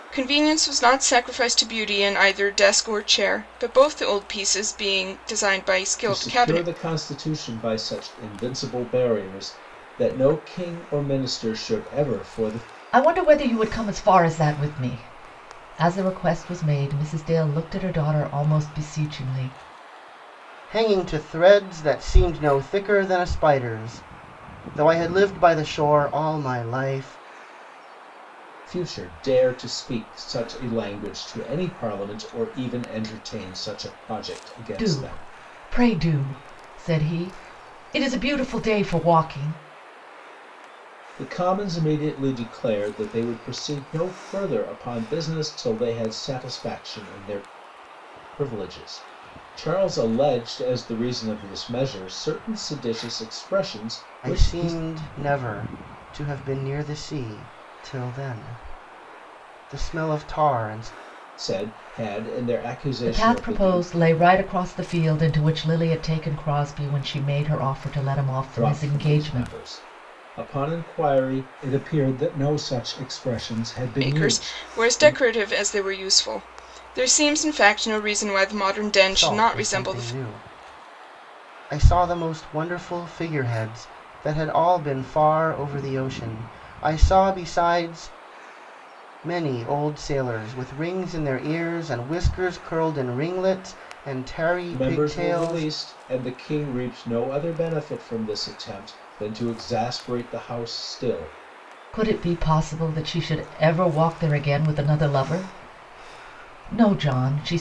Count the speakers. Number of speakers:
four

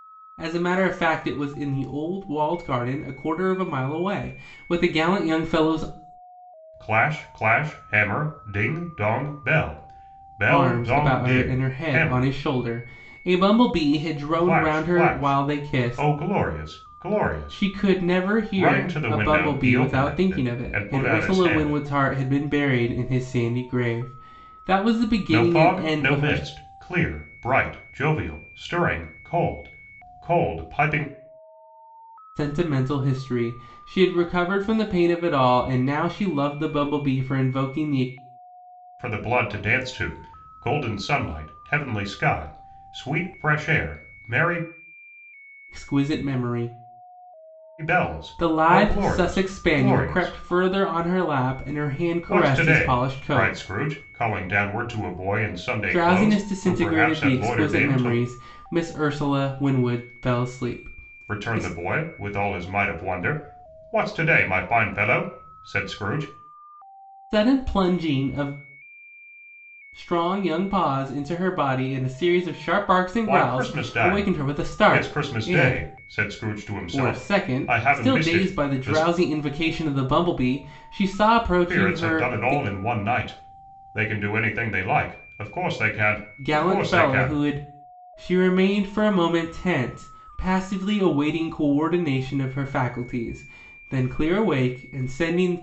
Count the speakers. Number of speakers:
two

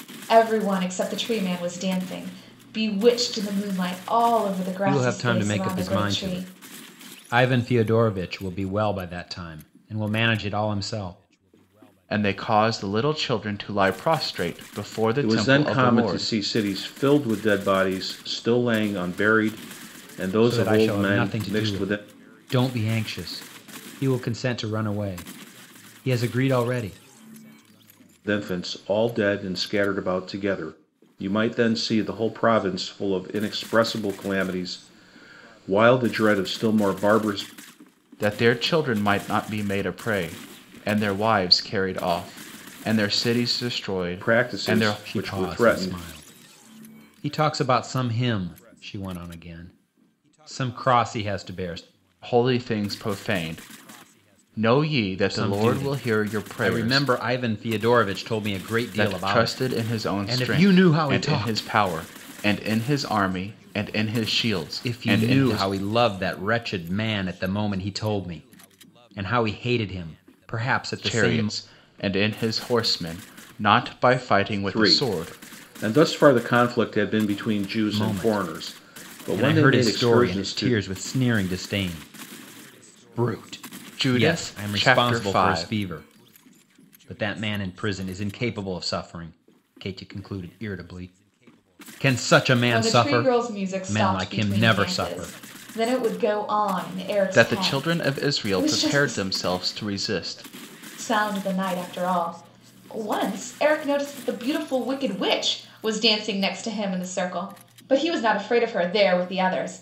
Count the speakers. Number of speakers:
four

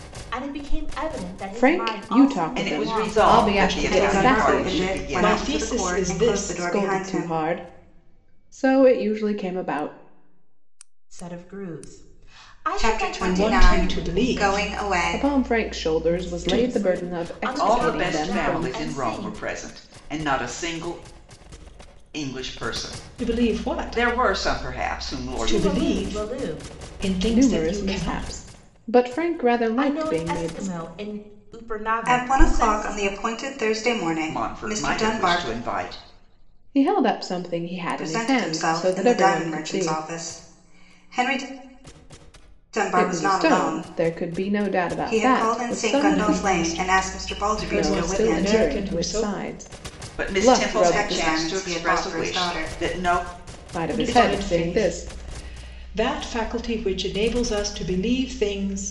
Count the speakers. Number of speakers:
five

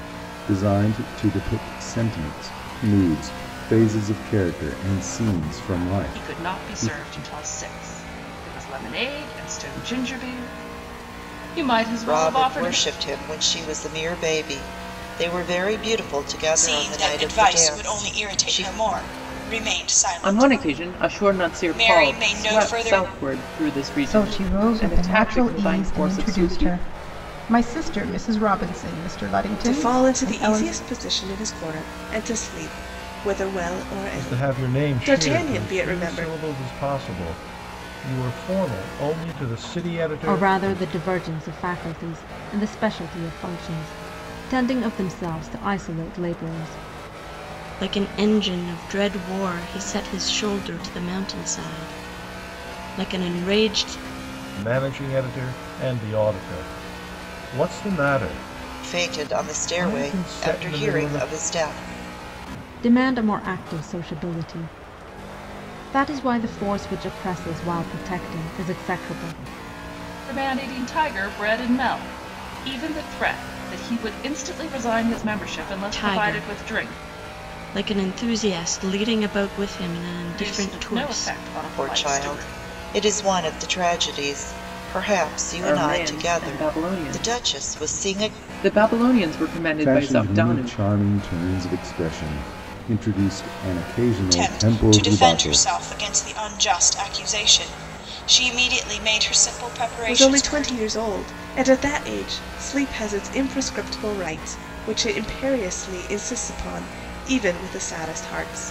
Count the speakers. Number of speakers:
ten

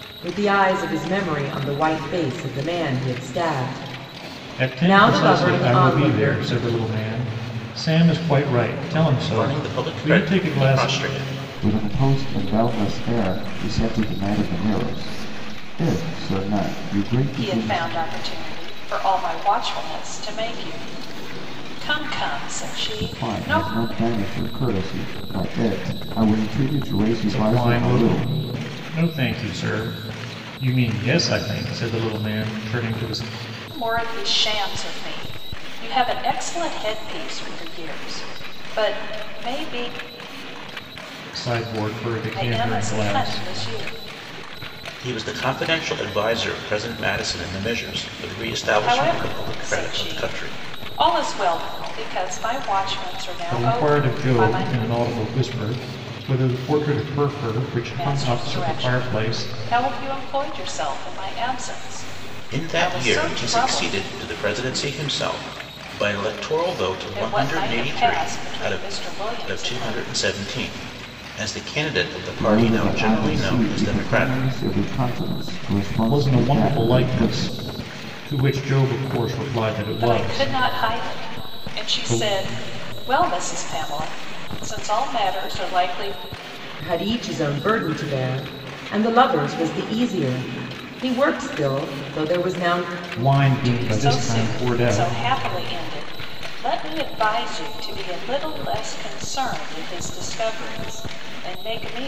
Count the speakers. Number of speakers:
five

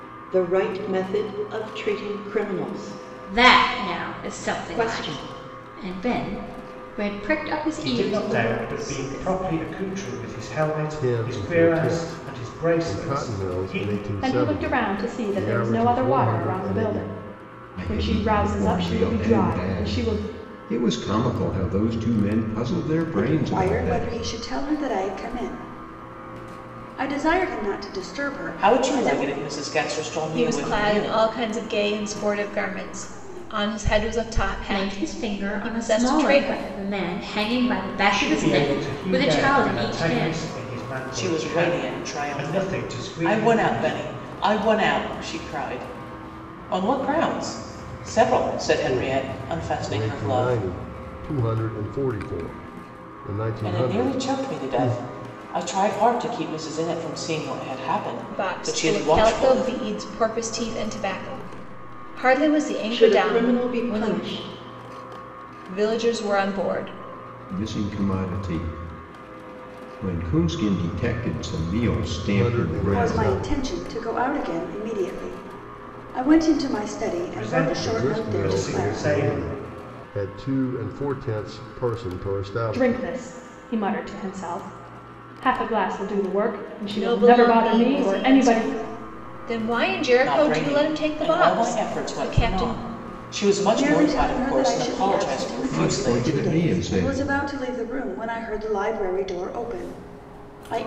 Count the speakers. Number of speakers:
nine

